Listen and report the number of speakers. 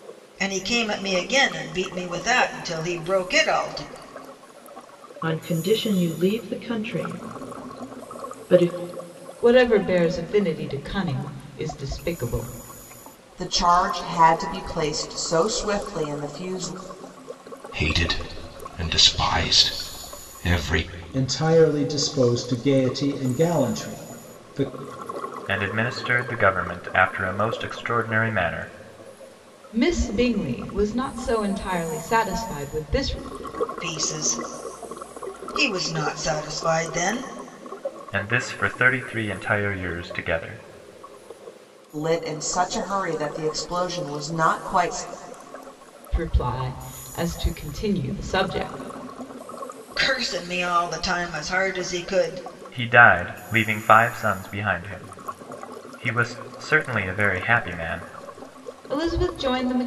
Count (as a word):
seven